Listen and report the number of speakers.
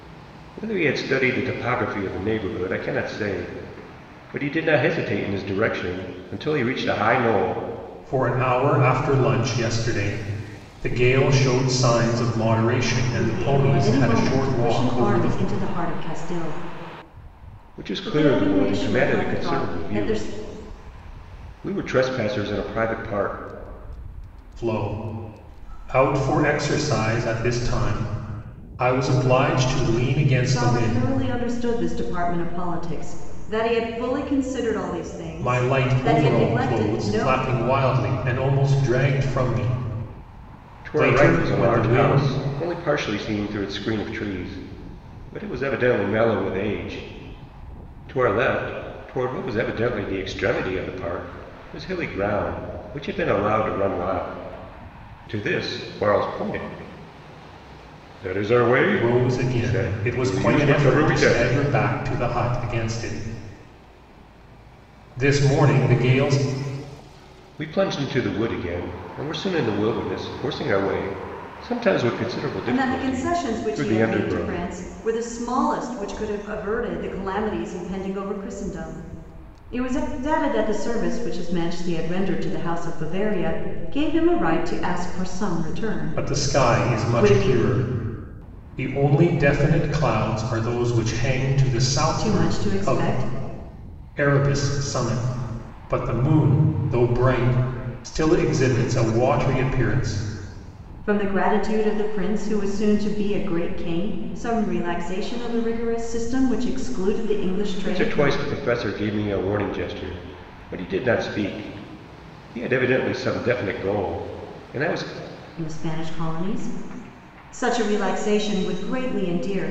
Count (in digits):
3